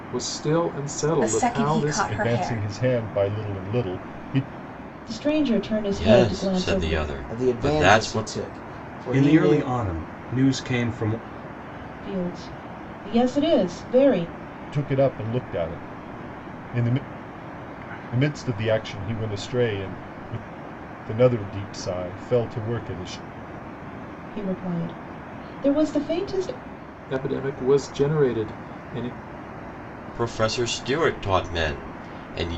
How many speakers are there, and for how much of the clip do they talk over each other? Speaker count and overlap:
seven, about 13%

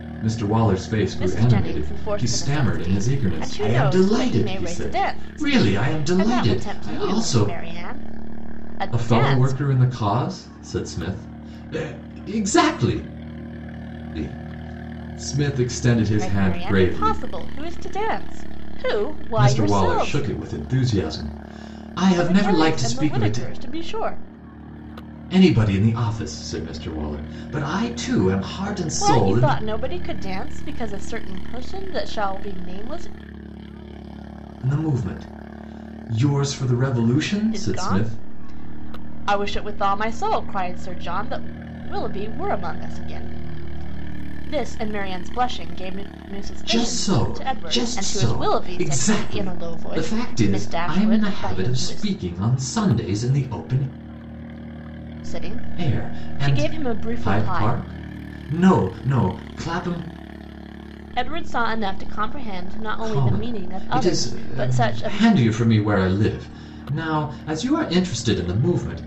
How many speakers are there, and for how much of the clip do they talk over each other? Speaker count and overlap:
two, about 31%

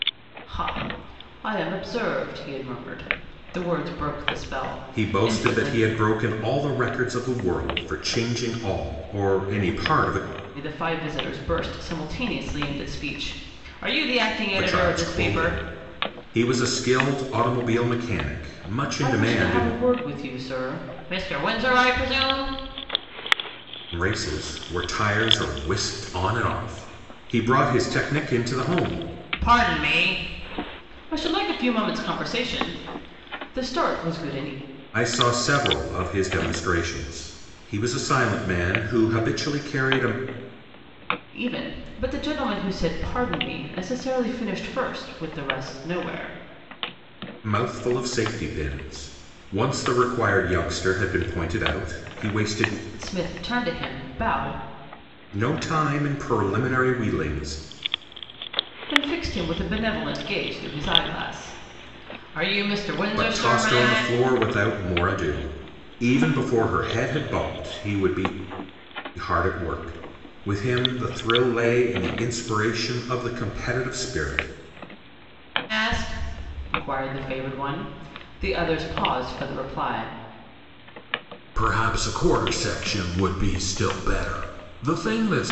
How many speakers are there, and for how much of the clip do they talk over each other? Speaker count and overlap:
two, about 5%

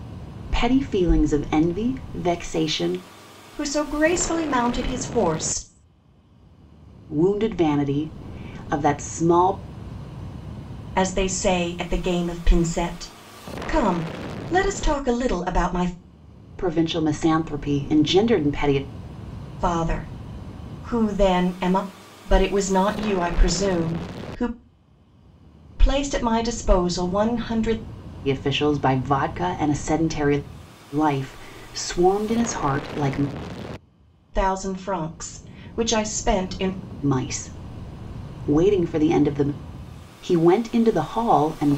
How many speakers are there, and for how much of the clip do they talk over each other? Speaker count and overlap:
two, no overlap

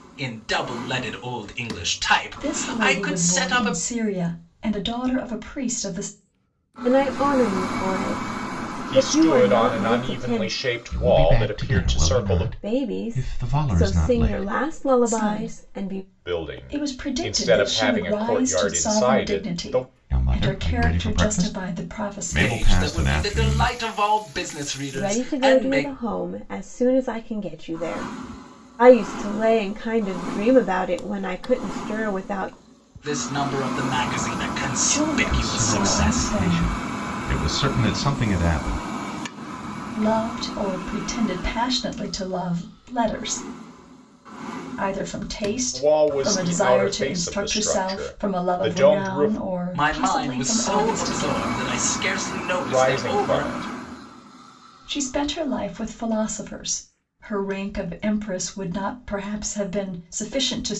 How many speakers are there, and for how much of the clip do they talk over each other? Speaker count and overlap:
five, about 41%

